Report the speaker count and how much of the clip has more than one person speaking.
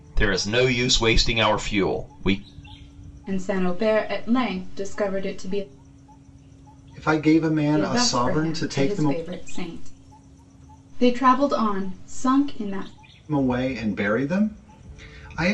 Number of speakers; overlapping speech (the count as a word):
three, about 9%